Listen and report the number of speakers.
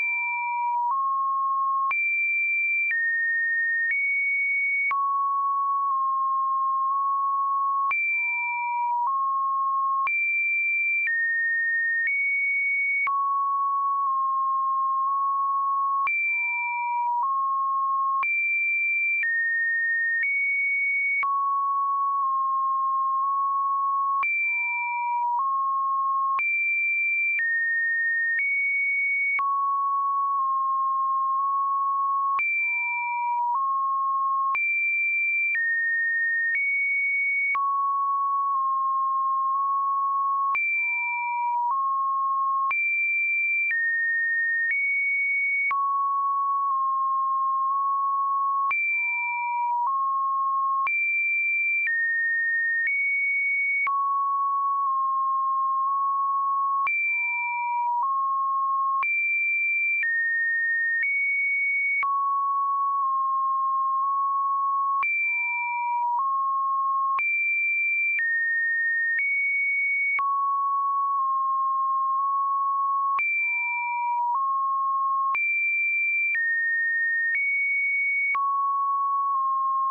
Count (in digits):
0